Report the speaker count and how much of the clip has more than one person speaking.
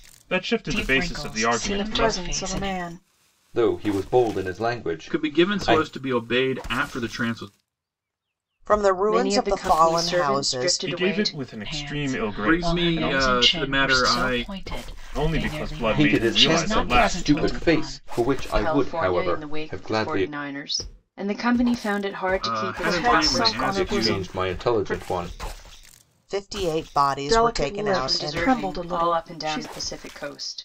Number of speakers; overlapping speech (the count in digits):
7, about 60%